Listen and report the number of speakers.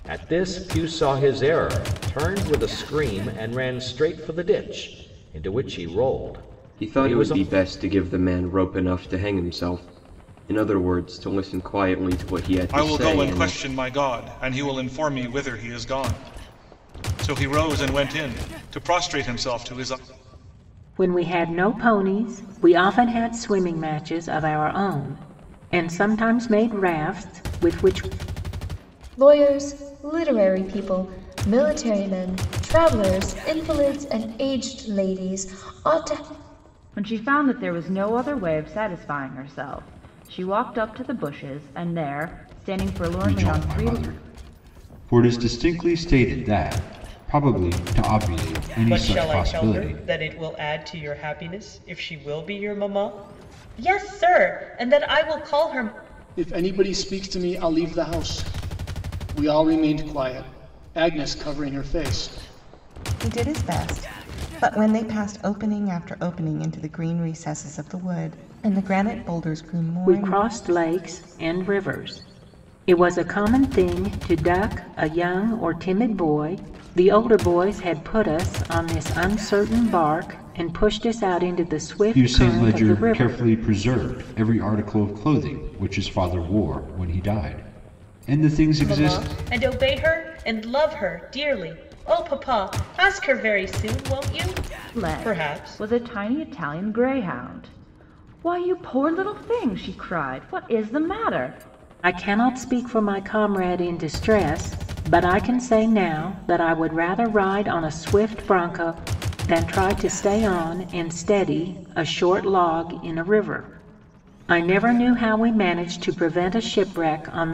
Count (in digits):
10